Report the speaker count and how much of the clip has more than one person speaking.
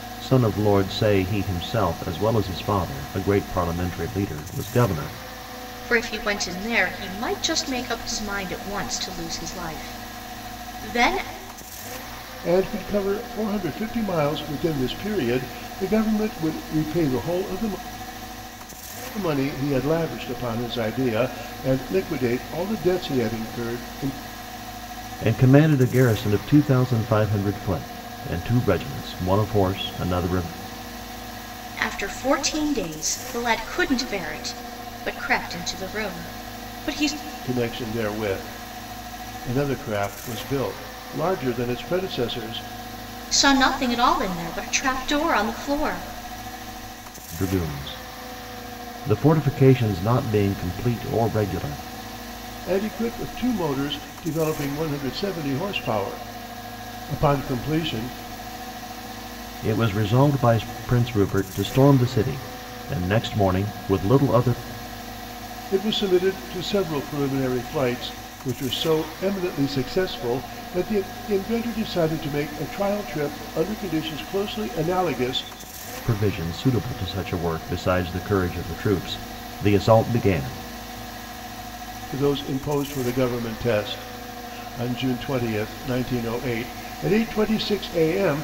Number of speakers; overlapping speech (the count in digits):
3, no overlap